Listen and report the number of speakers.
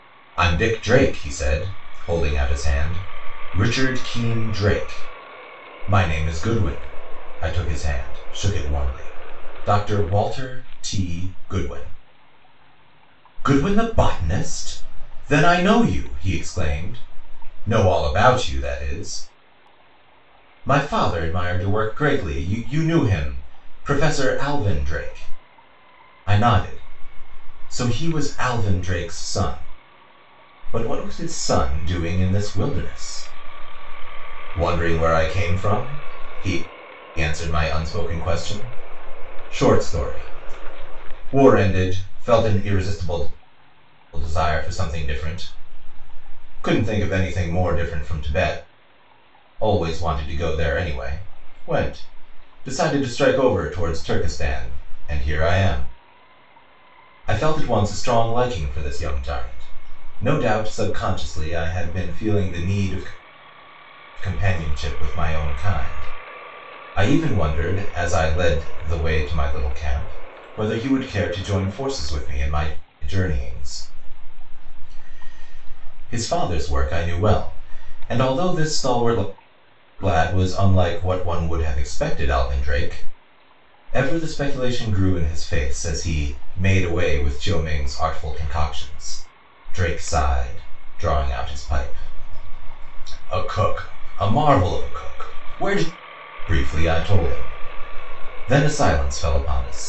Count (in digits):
1